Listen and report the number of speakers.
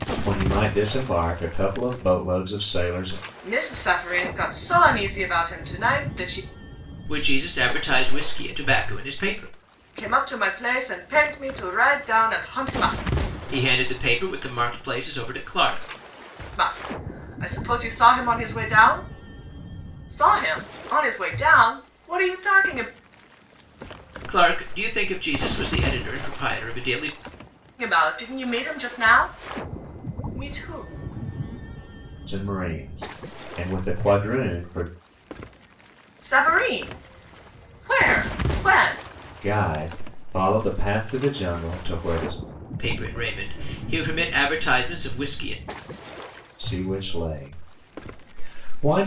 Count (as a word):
three